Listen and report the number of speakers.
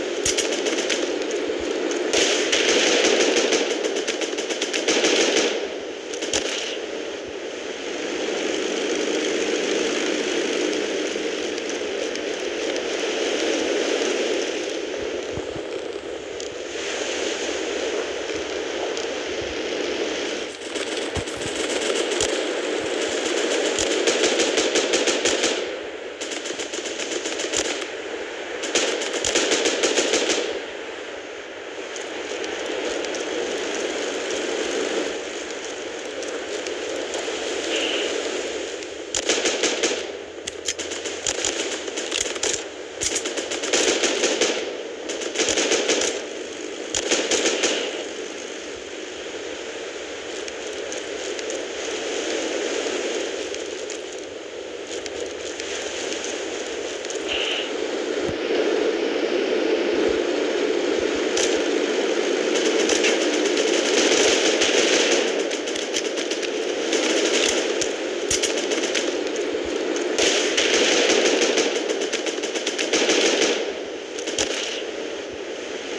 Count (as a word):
zero